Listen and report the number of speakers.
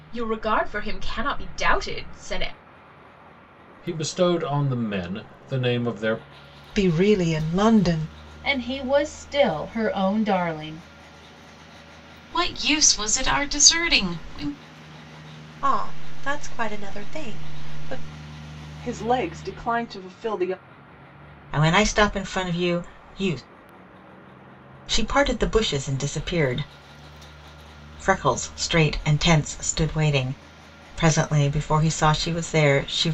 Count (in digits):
8